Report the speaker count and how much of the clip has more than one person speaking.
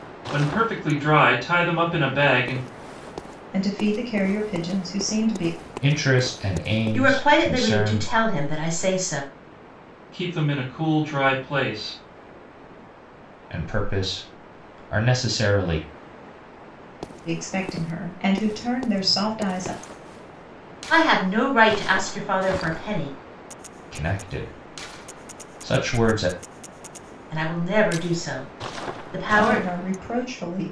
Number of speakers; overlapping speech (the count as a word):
four, about 5%